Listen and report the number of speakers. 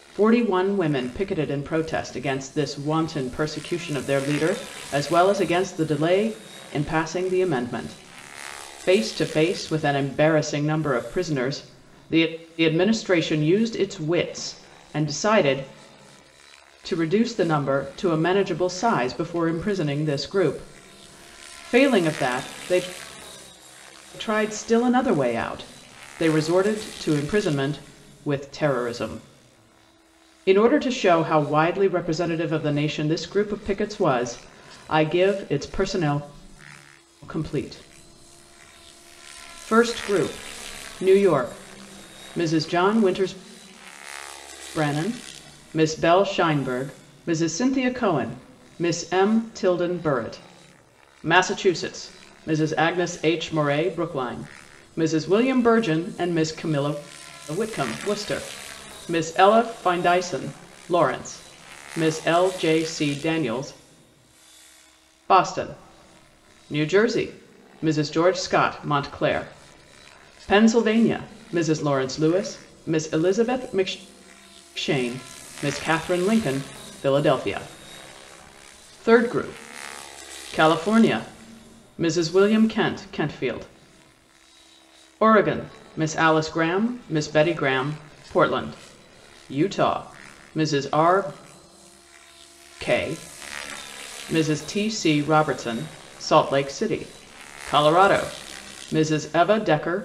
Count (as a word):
one